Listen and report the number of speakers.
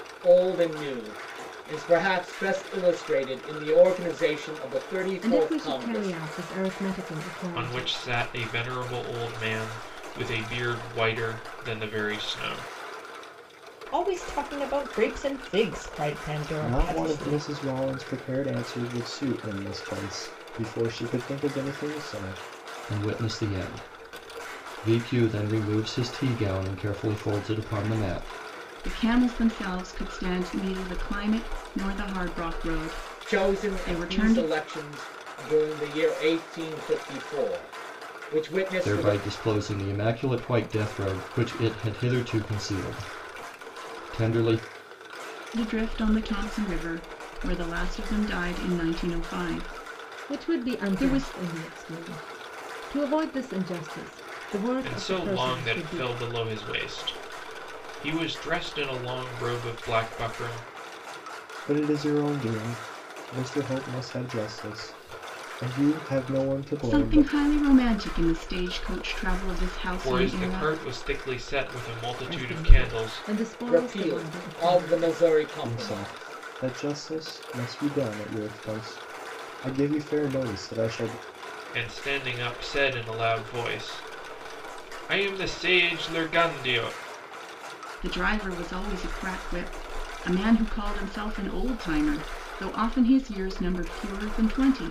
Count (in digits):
7